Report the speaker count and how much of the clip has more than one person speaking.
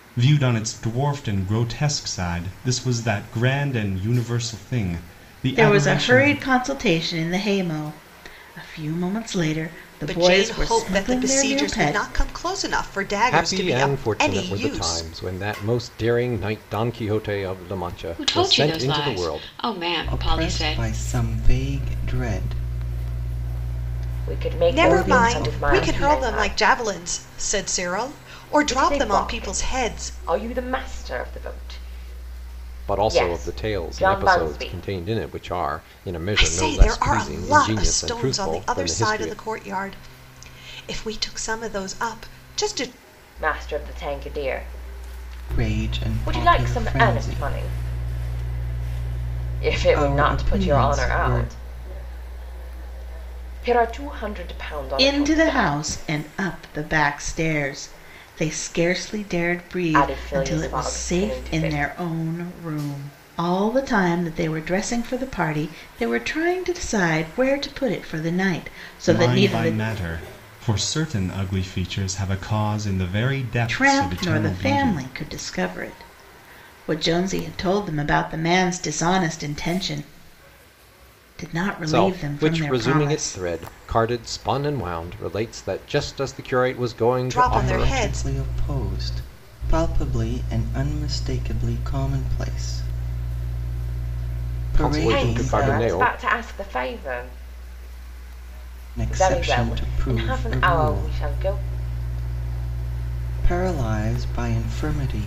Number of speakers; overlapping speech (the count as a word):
seven, about 30%